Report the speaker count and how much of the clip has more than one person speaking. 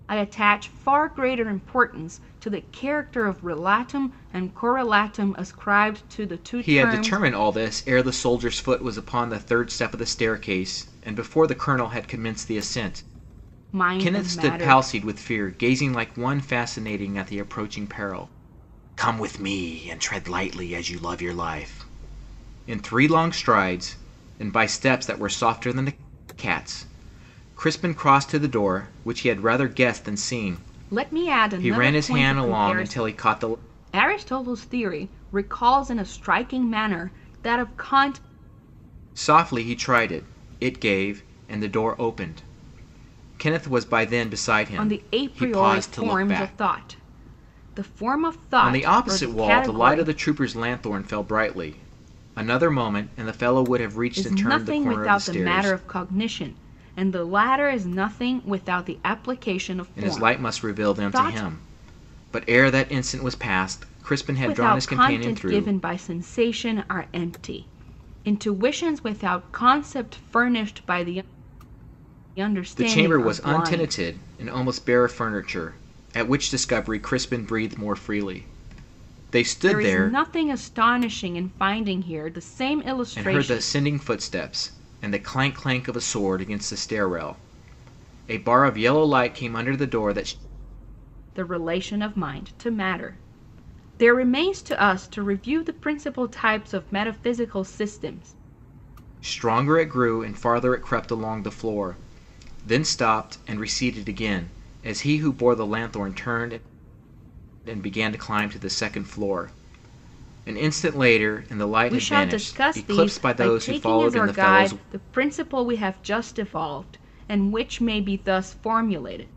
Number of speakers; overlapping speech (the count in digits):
2, about 15%